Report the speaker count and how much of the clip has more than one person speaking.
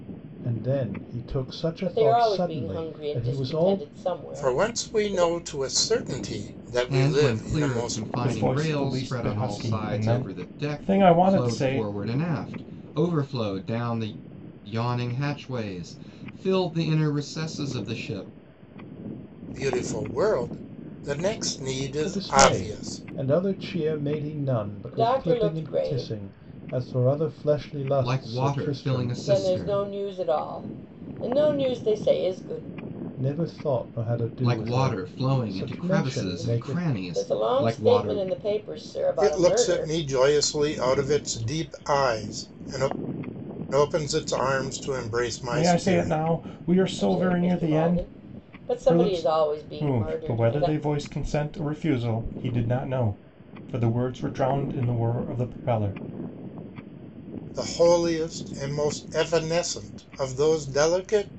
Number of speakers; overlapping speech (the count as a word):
five, about 34%